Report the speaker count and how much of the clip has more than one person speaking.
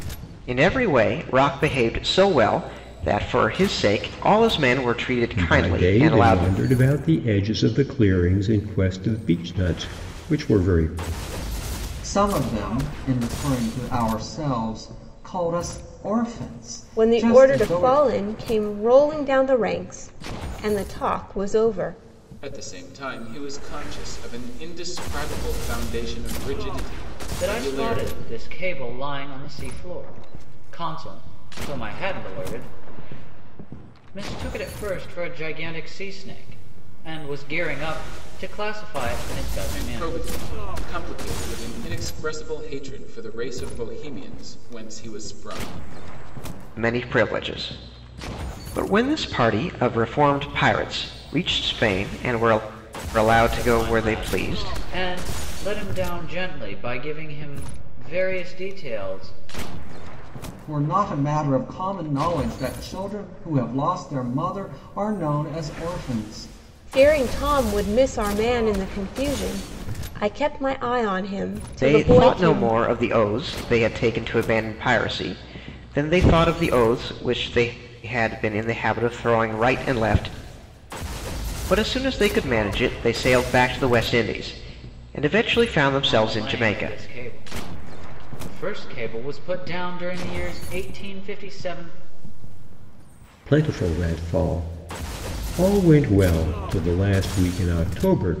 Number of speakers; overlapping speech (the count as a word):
six, about 7%